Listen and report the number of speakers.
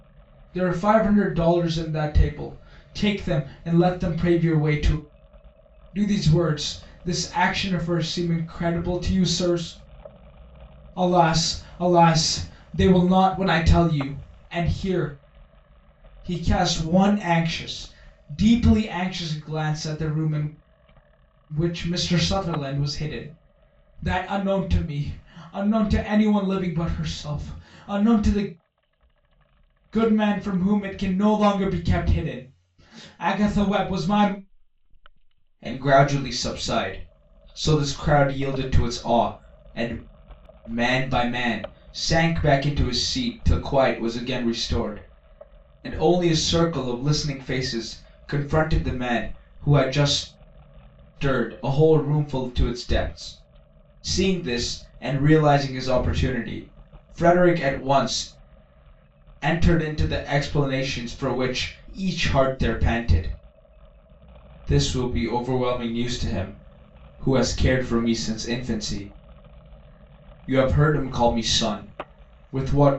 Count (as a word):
one